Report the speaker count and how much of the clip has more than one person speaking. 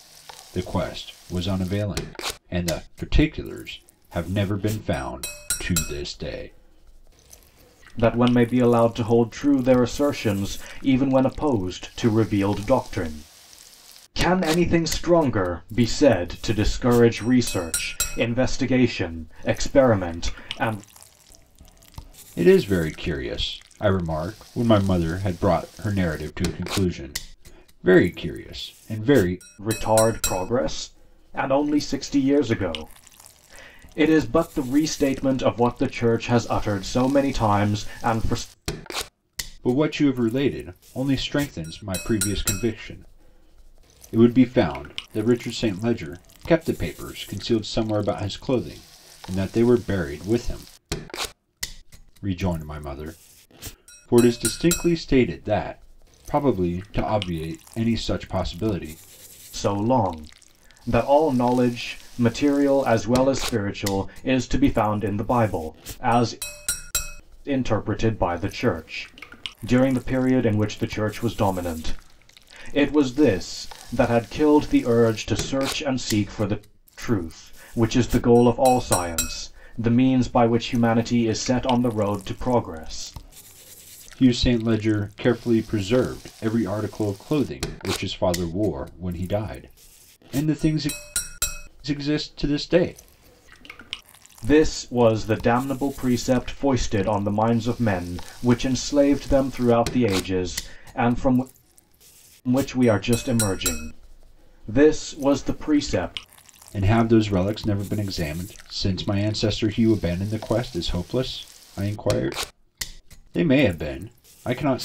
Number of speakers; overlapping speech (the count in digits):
2, no overlap